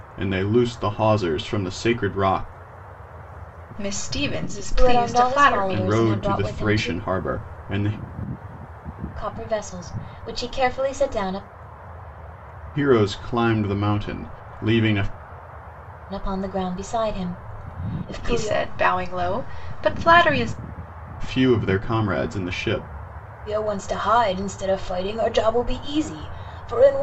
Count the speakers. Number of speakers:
3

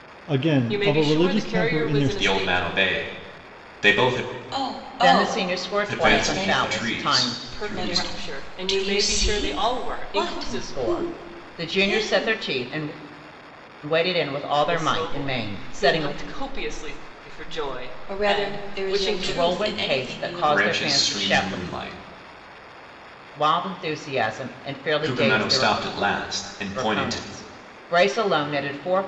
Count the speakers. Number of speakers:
5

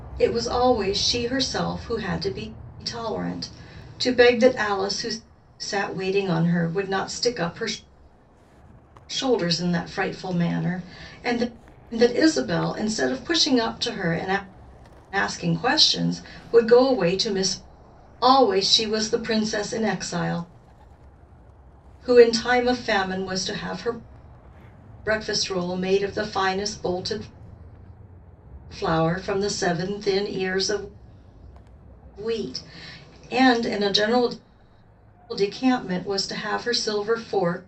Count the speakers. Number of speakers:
1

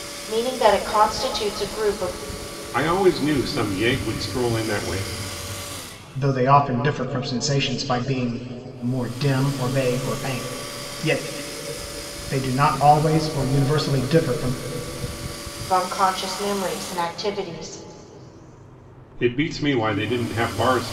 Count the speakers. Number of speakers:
3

